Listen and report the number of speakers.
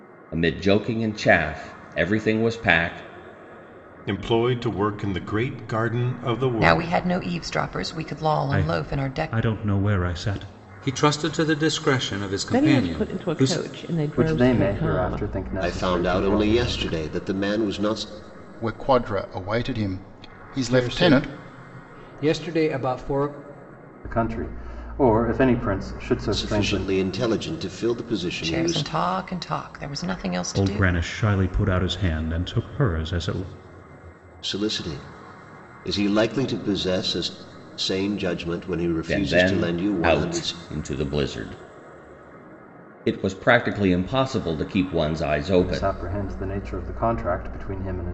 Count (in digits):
10